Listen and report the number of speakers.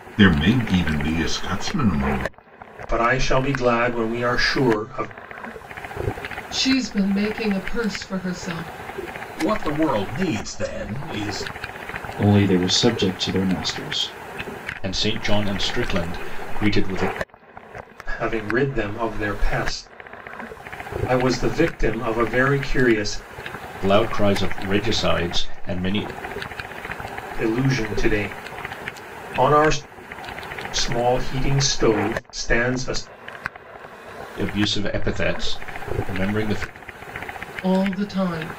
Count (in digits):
6